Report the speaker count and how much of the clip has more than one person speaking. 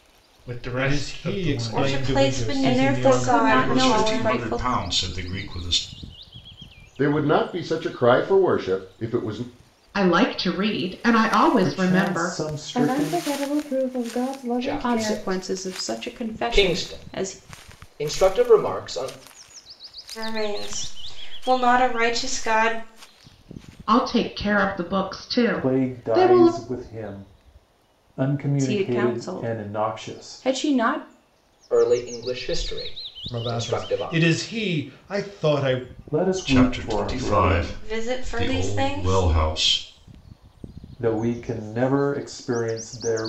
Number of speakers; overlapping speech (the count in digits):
10, about 31%